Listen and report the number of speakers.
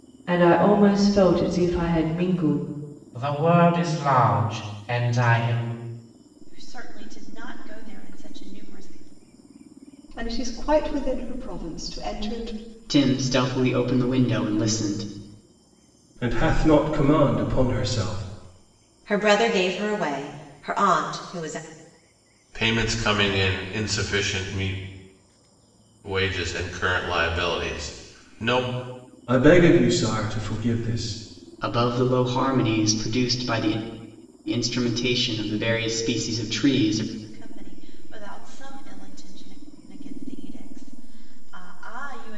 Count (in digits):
8